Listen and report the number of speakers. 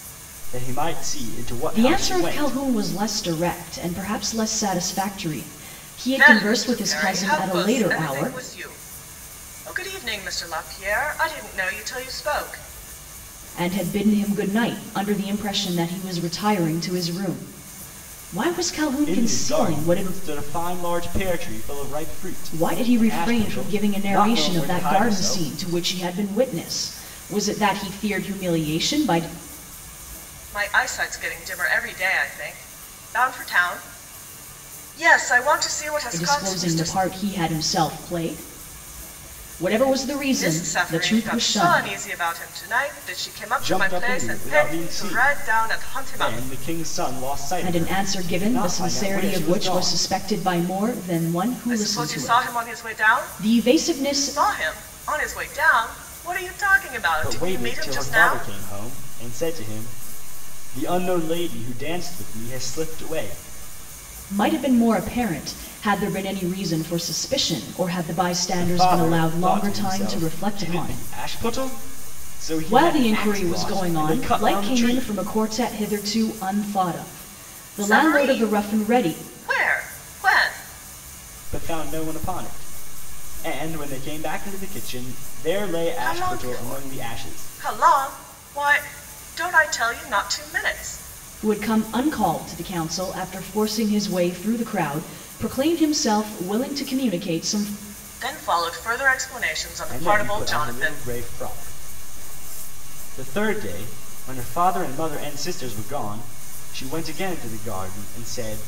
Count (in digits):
3